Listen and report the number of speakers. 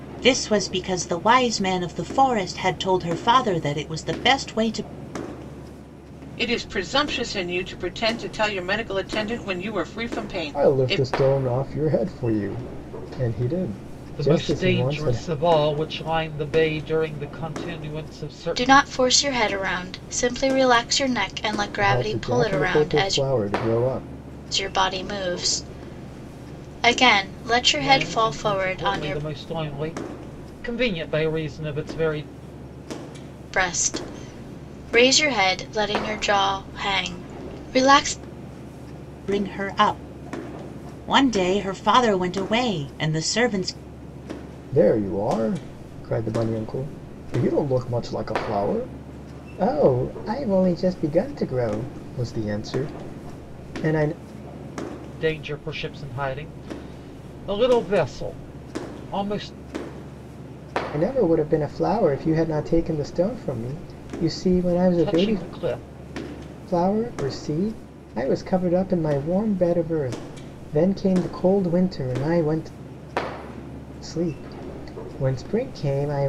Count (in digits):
5